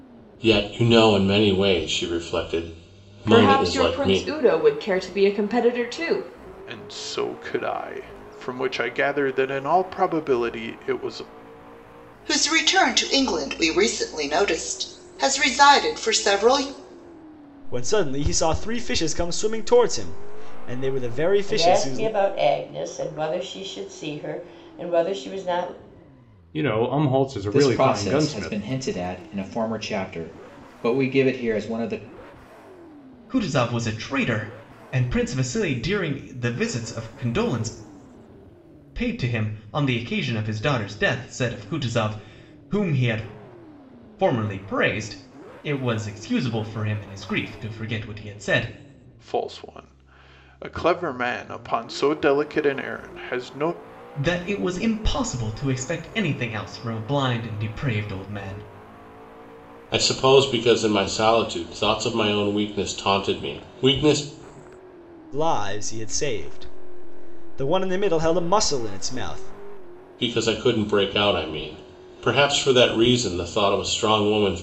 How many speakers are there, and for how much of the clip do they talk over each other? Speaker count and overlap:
9, about 4%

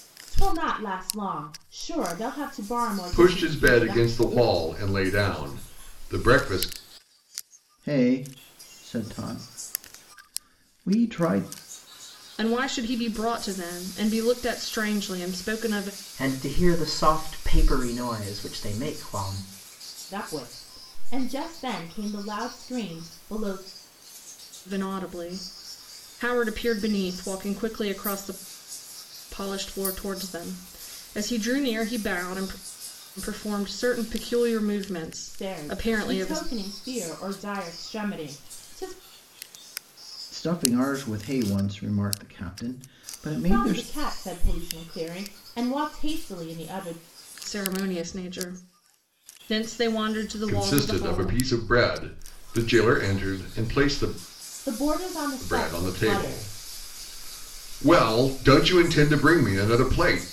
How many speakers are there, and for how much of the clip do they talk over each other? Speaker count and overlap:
5, about 8%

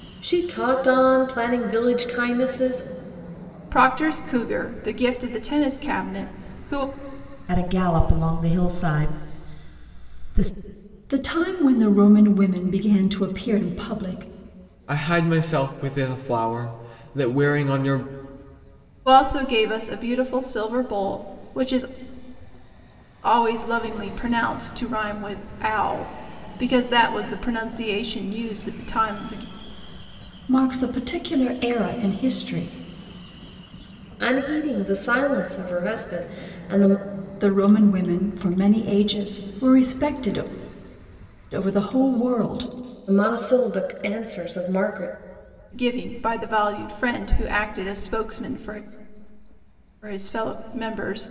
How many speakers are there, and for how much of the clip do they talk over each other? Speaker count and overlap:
5, no overlap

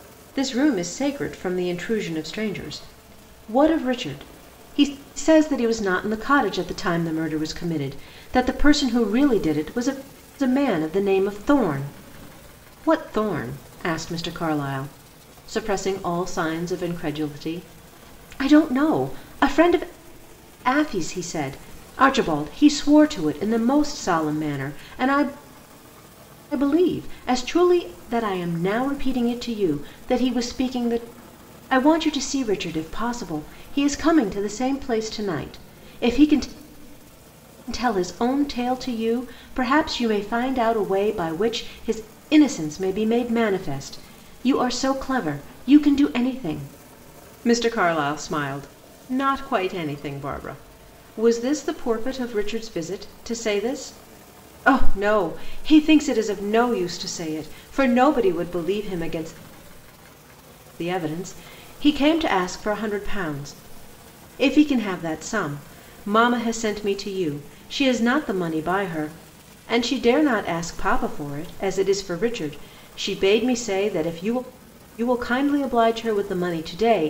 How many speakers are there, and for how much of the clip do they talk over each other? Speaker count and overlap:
1, no overlap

